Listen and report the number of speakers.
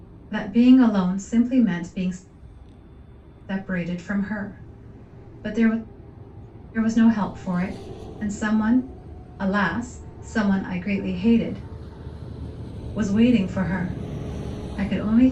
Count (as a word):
one